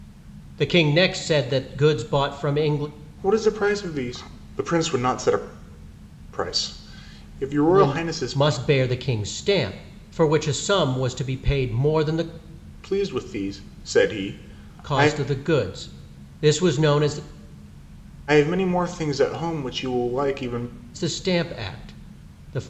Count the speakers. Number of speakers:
2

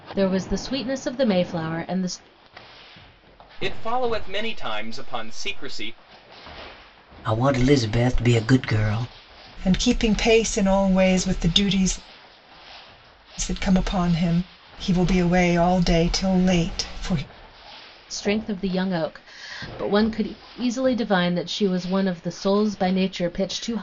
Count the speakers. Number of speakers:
4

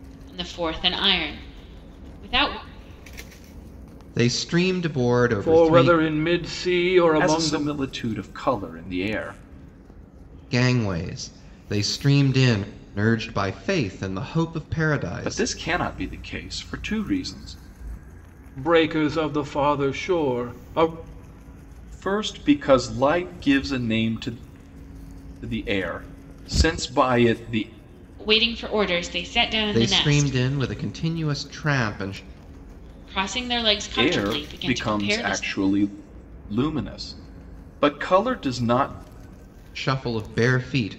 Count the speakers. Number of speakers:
4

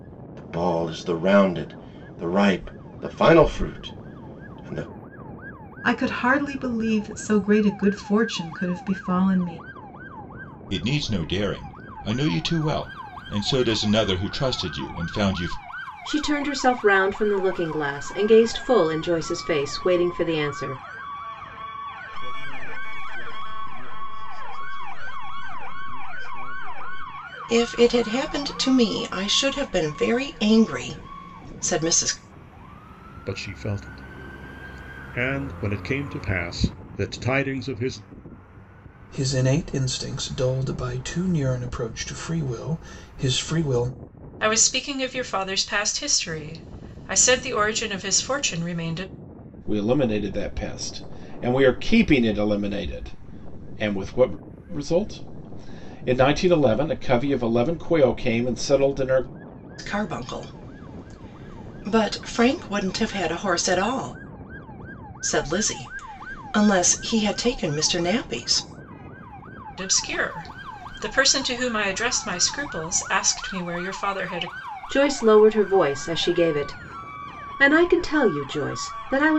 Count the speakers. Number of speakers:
10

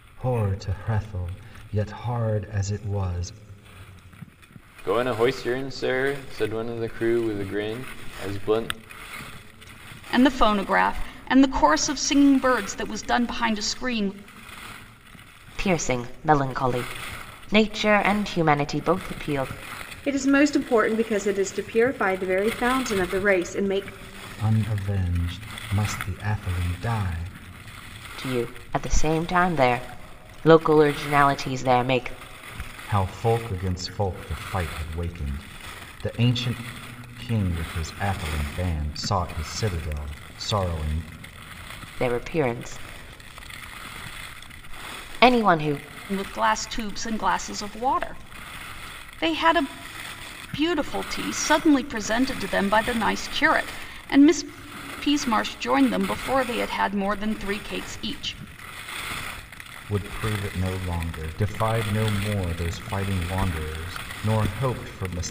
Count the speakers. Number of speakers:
5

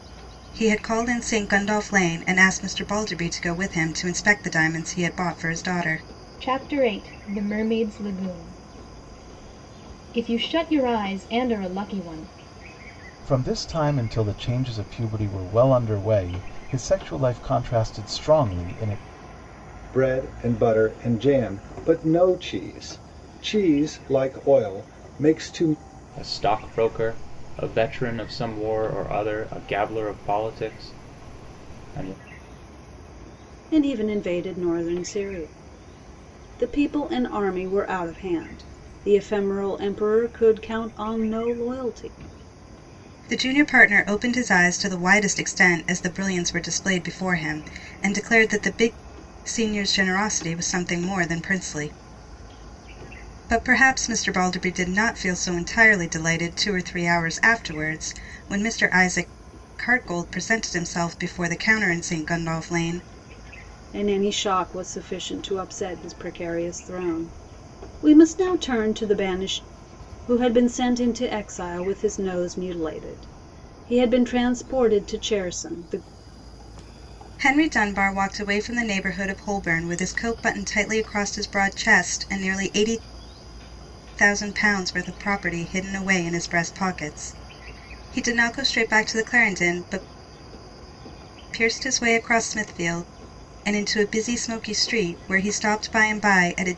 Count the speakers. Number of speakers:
6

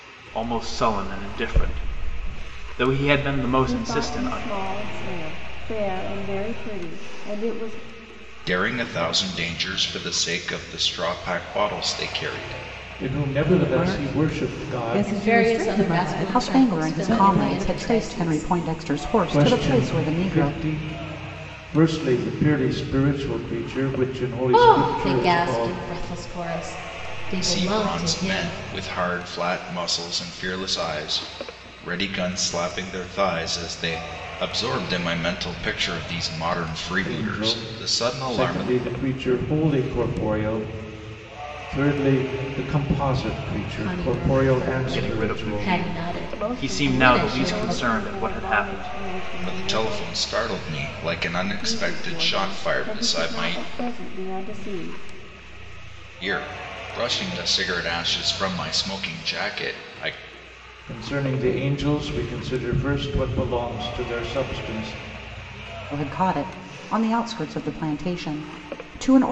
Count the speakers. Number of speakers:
7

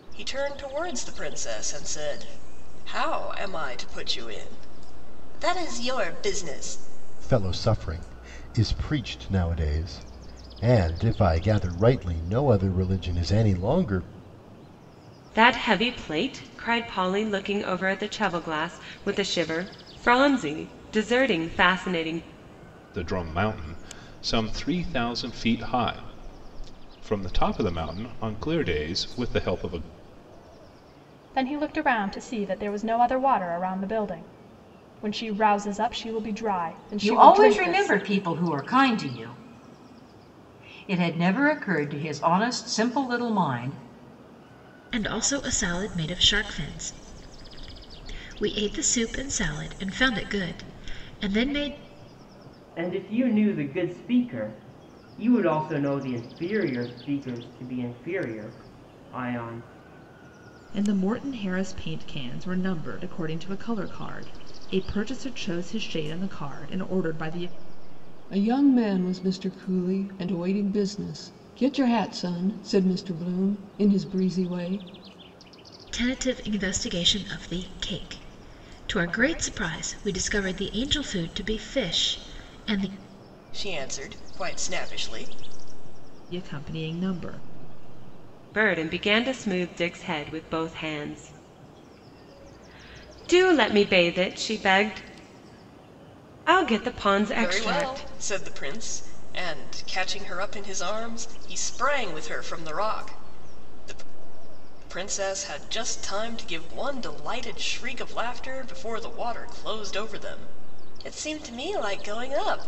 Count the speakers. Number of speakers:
10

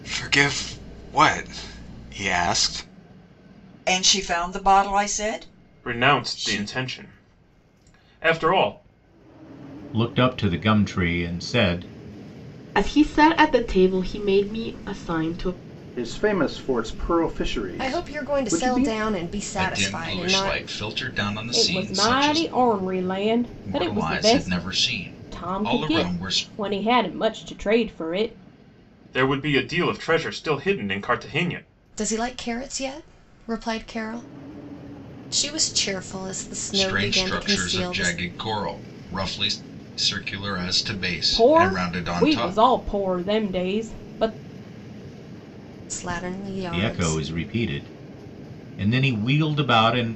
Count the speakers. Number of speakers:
9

